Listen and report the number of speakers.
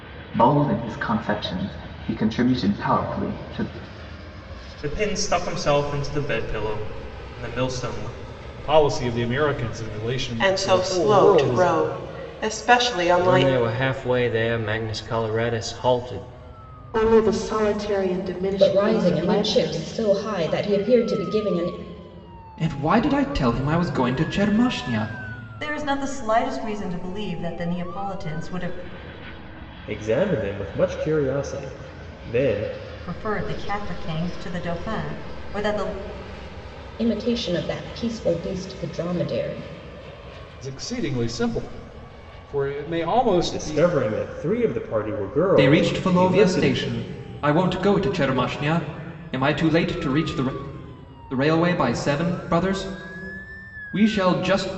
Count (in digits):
10